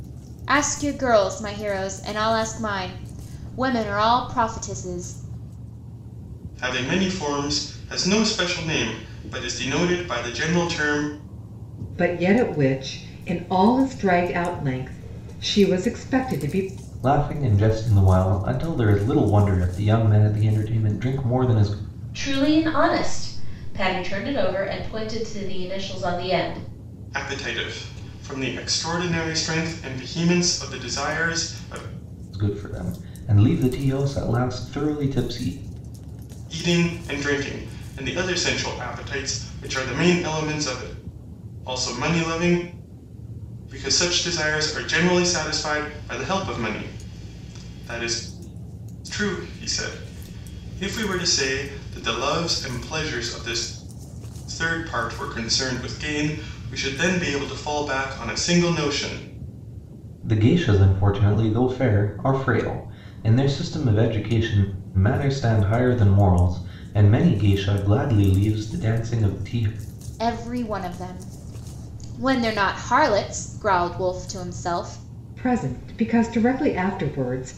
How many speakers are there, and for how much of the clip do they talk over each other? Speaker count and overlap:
5, no overlap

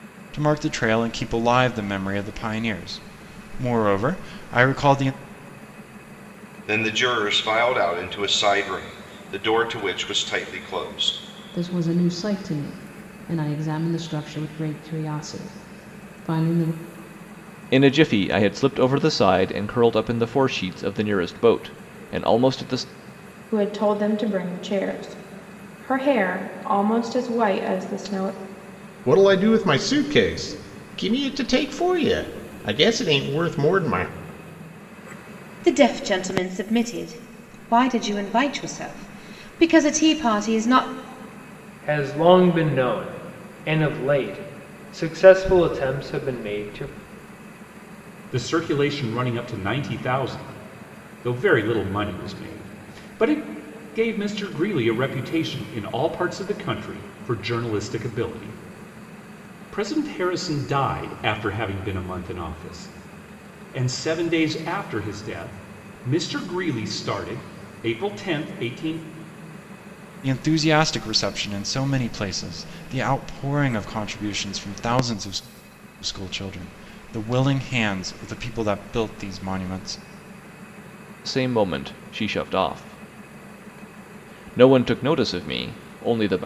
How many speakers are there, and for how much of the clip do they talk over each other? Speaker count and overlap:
9, no overlap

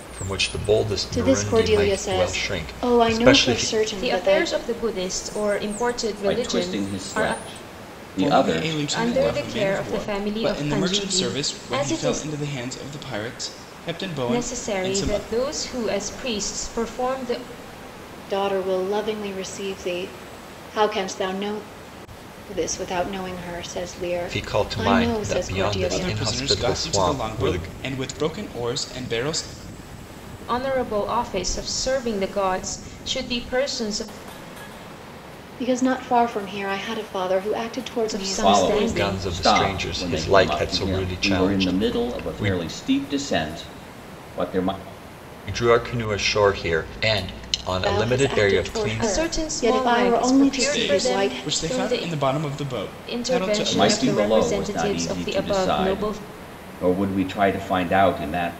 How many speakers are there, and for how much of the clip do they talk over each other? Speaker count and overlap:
5, about 43%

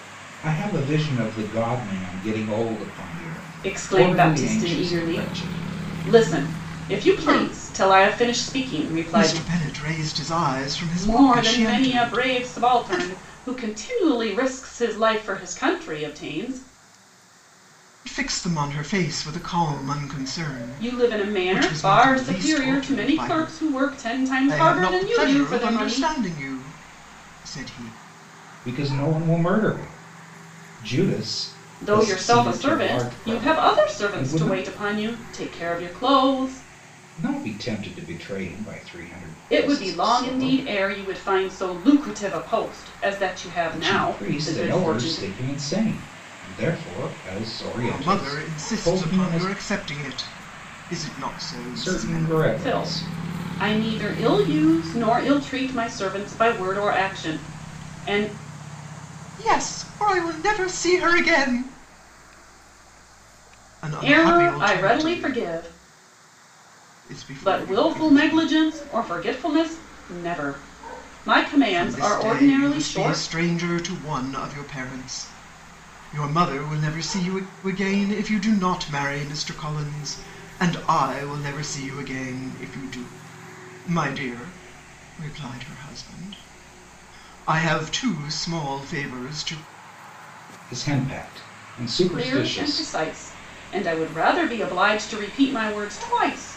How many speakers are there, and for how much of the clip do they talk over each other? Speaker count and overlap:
3, about 25%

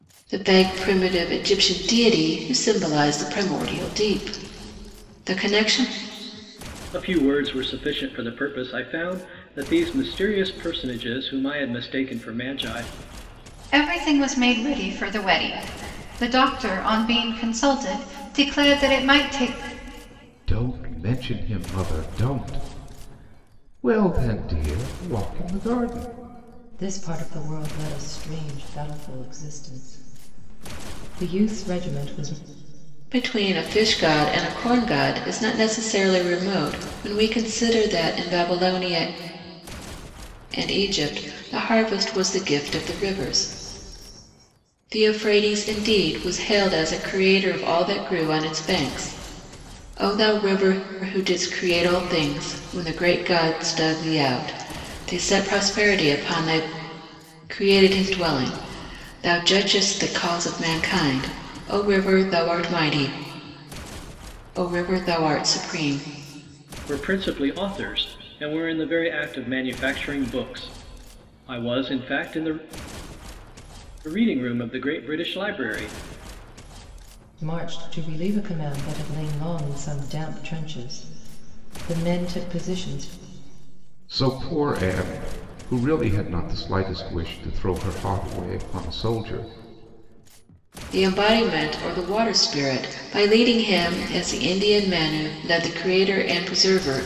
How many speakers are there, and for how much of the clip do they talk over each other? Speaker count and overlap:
5, no overlap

